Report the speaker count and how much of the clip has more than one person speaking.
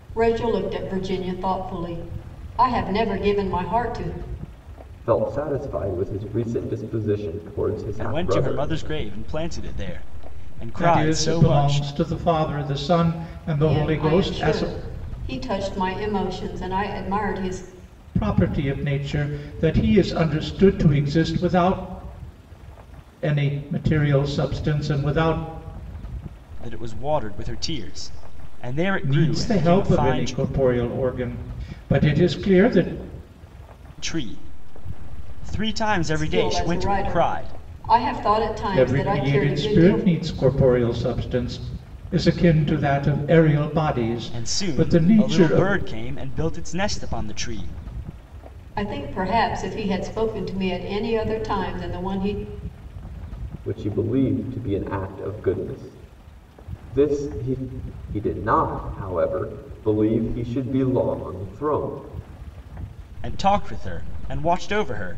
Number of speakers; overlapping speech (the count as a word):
four, about 13%